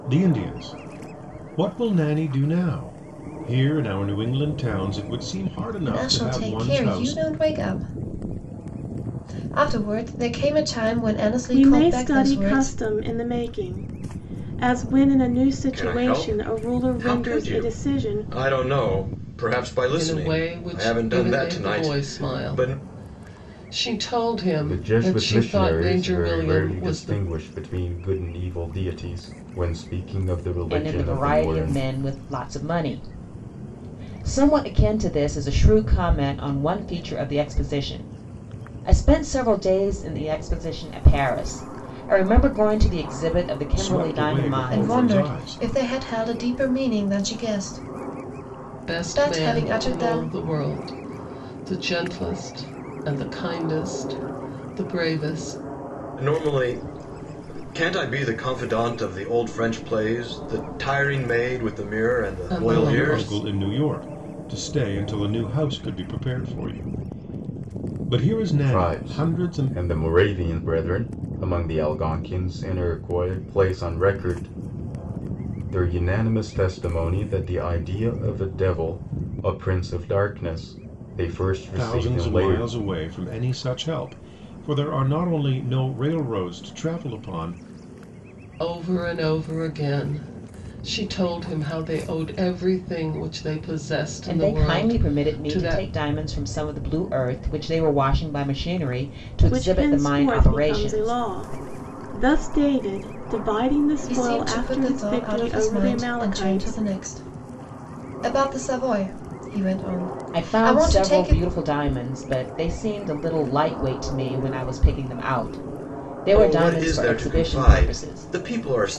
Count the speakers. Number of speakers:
seven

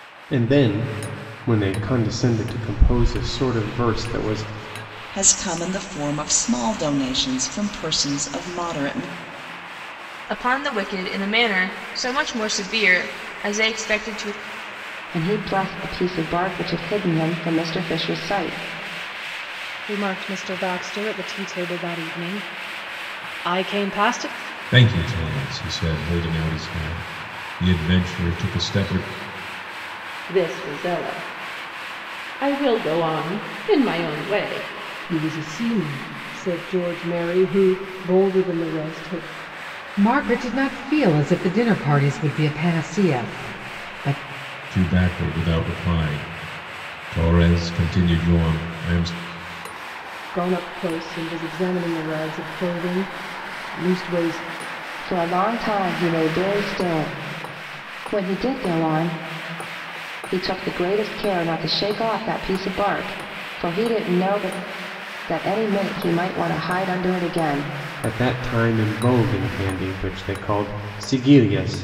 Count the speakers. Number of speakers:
nine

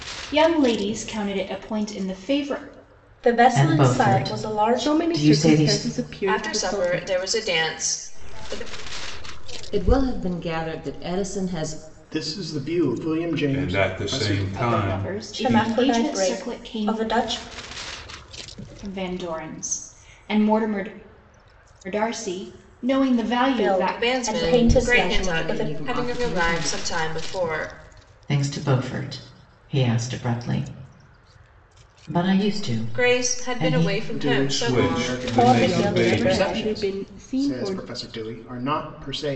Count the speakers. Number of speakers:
nine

